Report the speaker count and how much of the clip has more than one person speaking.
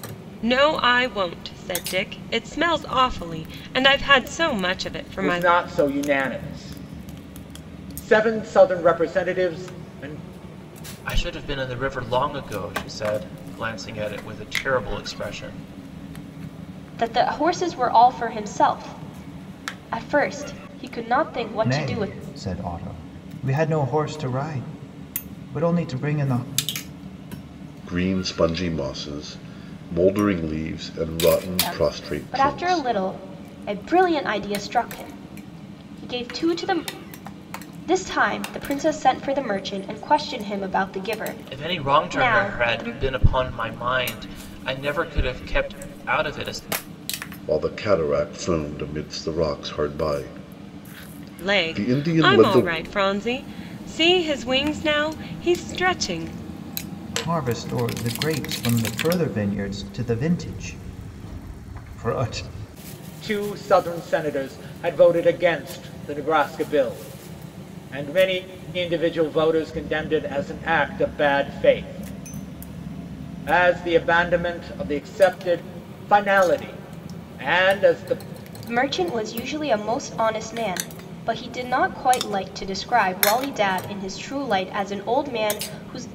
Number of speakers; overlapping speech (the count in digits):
6, about 6%